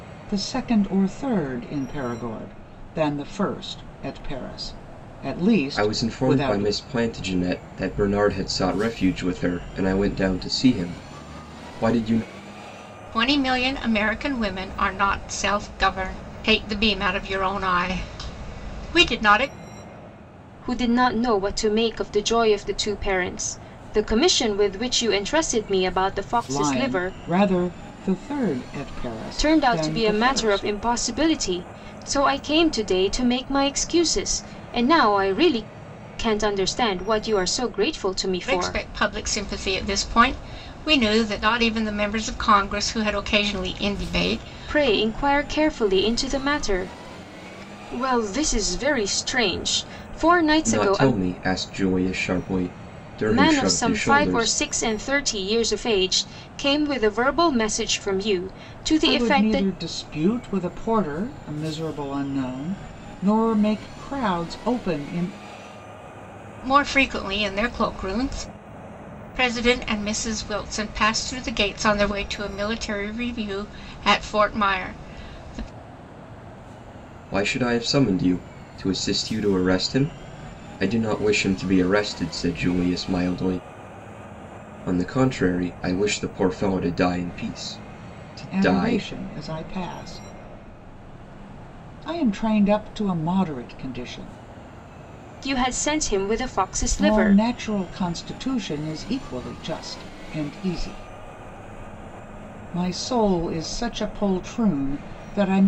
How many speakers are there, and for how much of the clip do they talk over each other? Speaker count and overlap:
4, about 7%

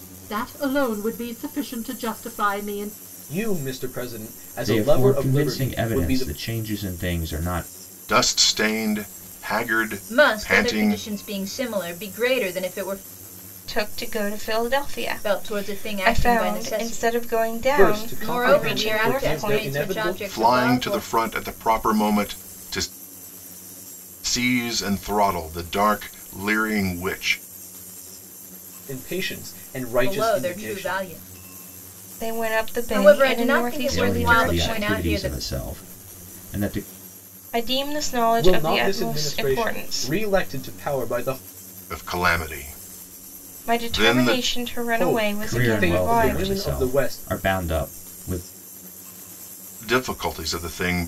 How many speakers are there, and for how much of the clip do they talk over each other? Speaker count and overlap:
6, about 33%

